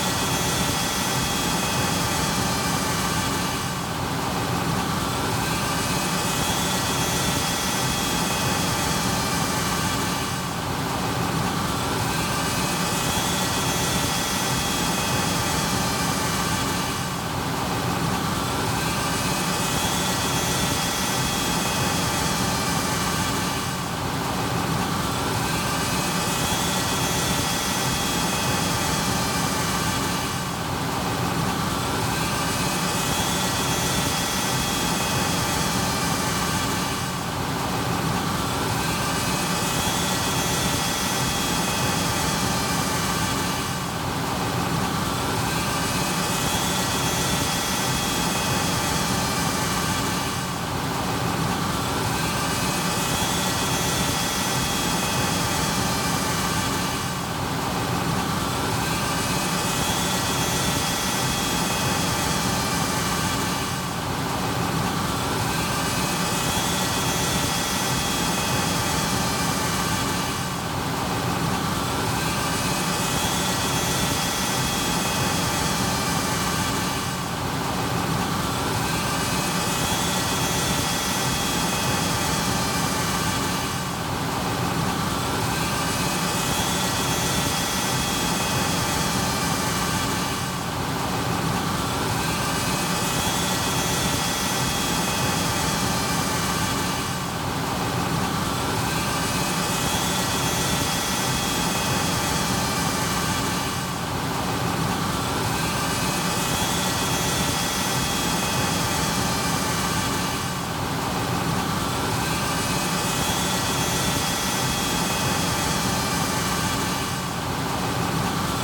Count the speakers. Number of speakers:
zero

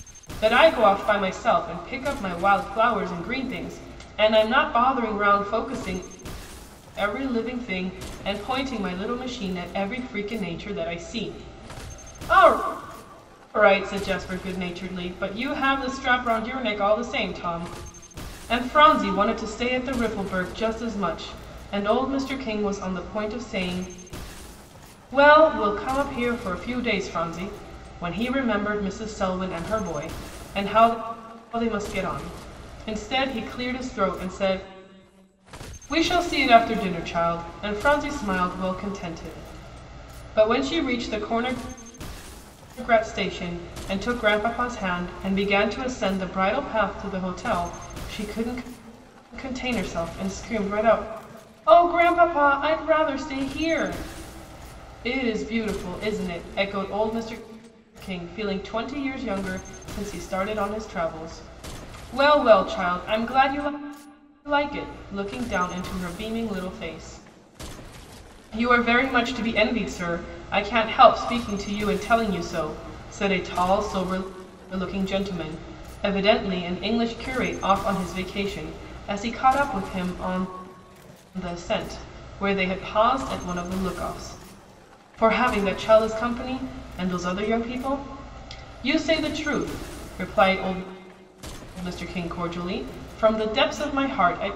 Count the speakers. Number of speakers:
one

